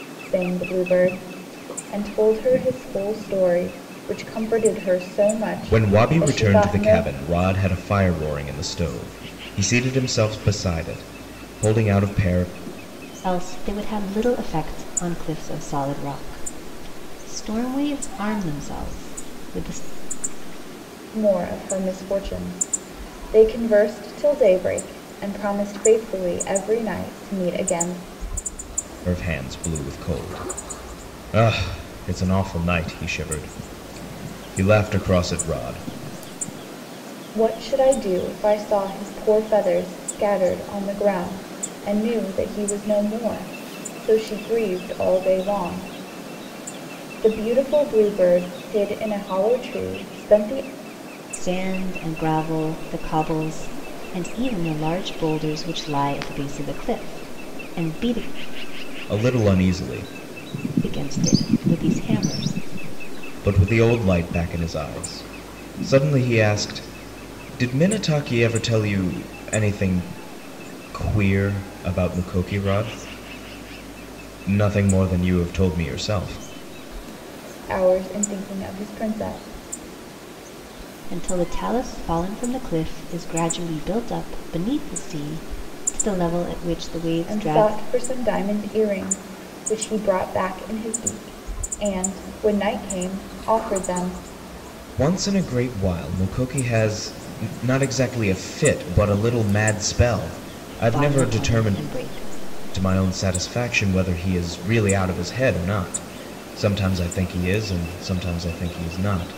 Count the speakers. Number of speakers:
3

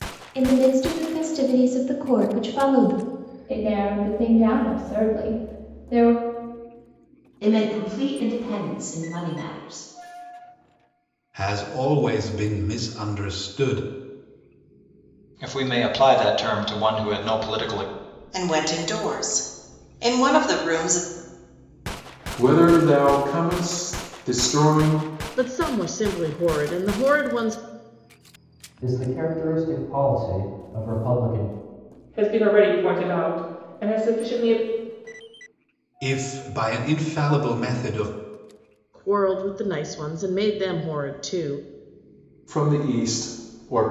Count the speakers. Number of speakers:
10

